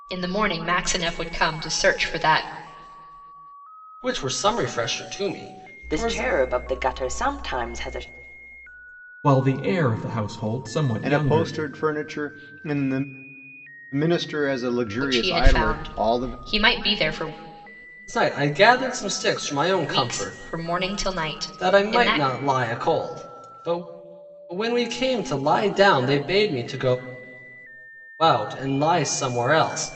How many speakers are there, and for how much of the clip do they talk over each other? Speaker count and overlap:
five, about 13%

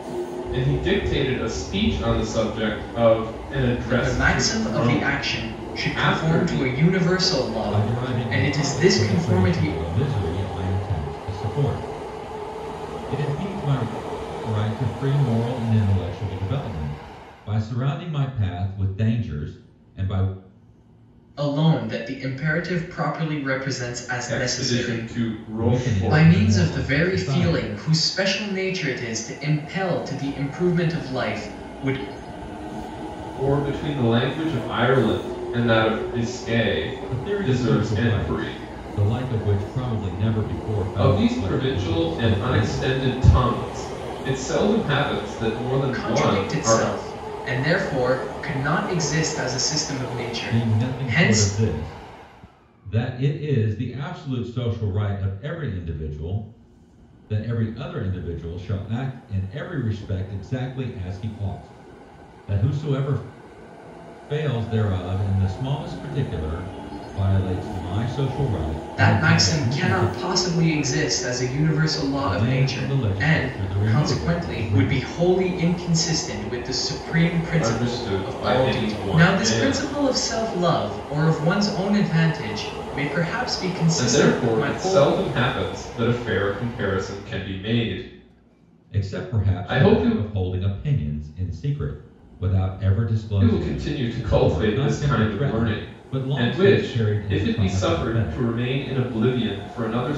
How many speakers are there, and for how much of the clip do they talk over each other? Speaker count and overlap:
three, about 27%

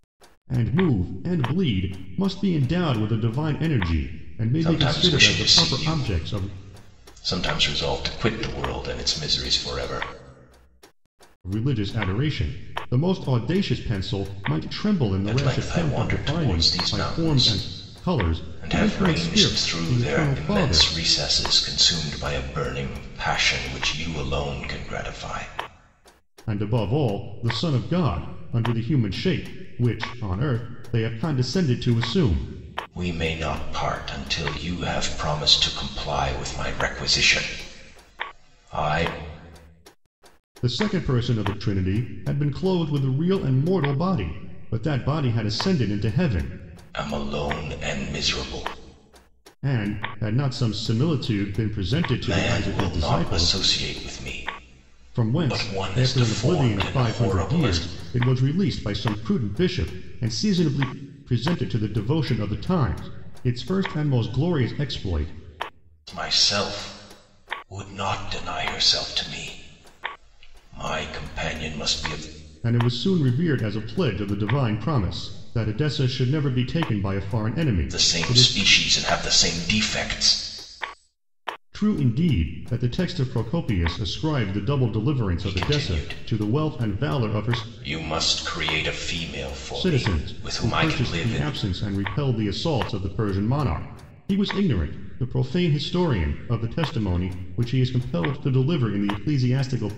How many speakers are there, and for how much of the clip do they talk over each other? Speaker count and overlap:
two, about 16%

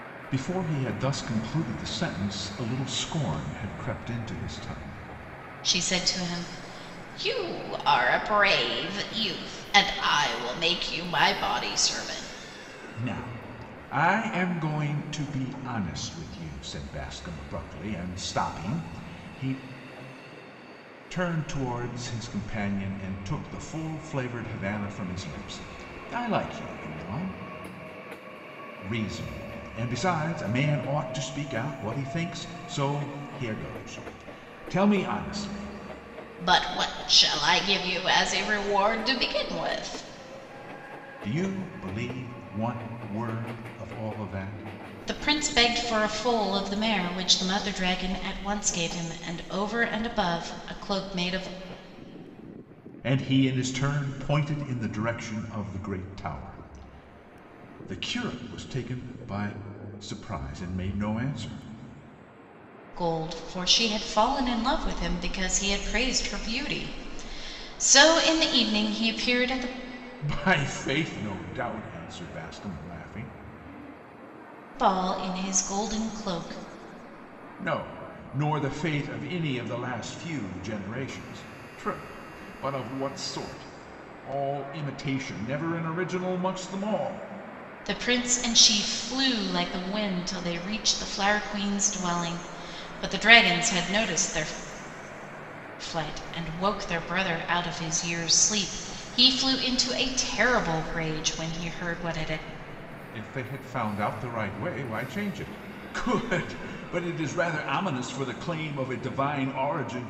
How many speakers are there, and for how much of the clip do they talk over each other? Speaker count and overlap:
two, no overlap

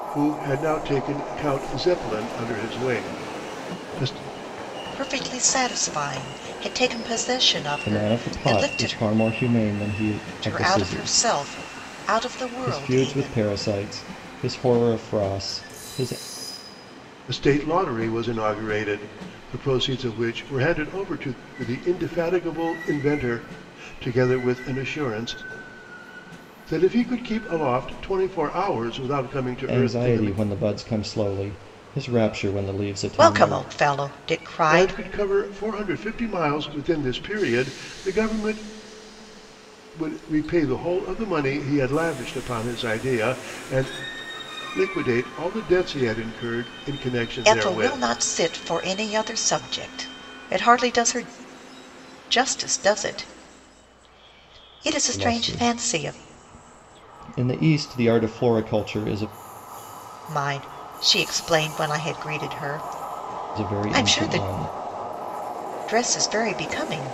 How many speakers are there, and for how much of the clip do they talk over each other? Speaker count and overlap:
three, about 11%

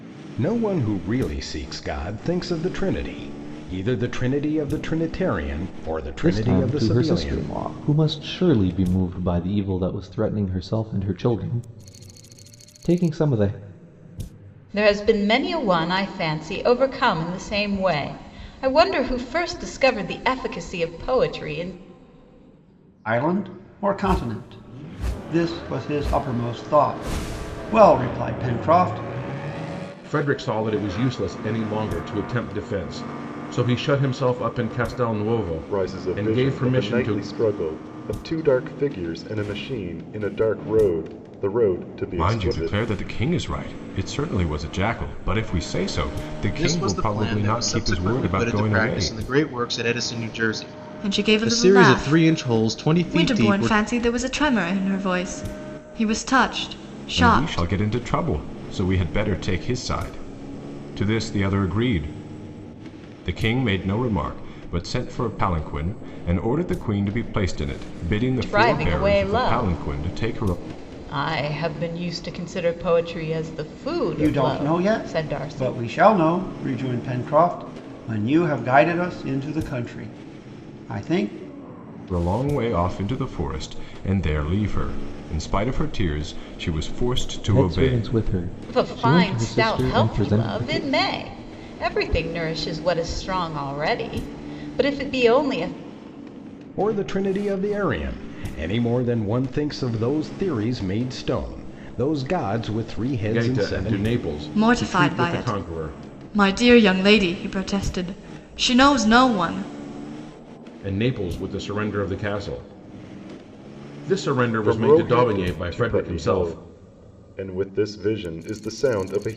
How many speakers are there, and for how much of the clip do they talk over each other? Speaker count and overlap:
nine, about 18%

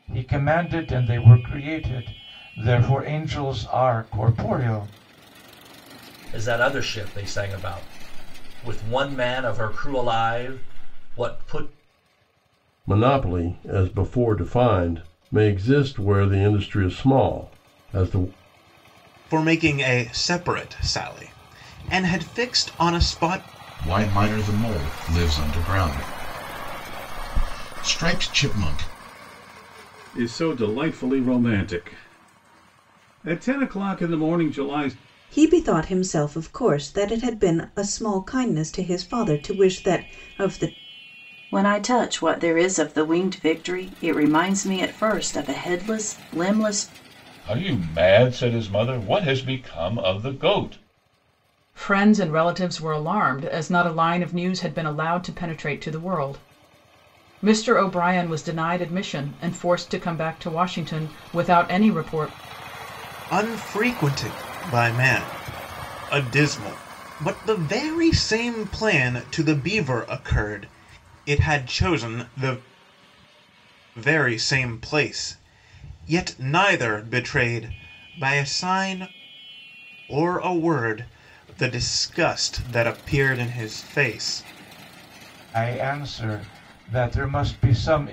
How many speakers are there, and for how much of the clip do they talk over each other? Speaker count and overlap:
ten, no overlap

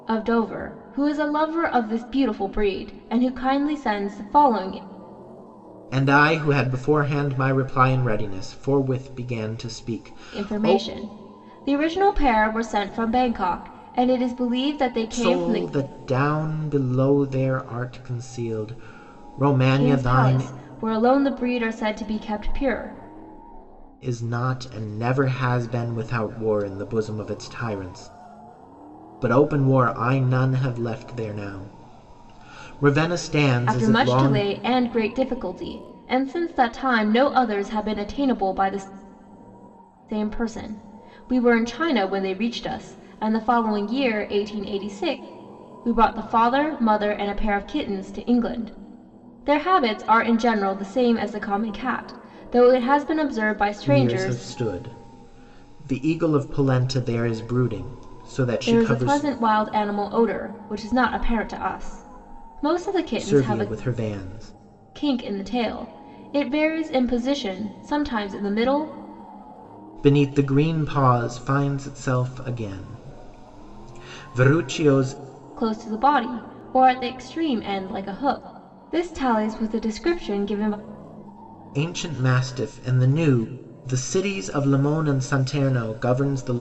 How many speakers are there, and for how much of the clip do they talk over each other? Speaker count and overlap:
two, about 5%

